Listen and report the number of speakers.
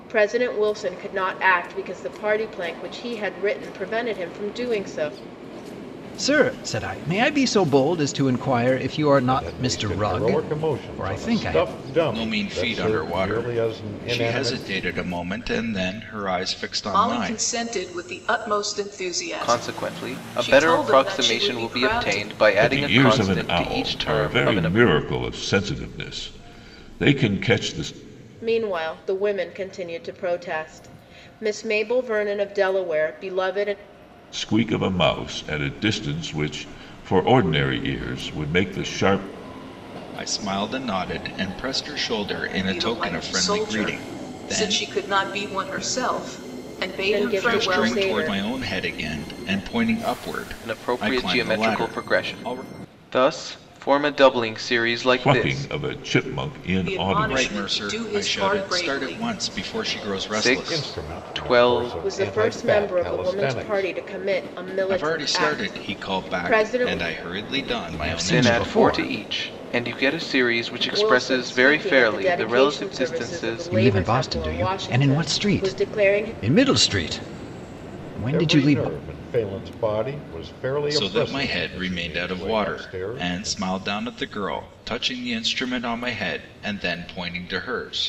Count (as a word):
seven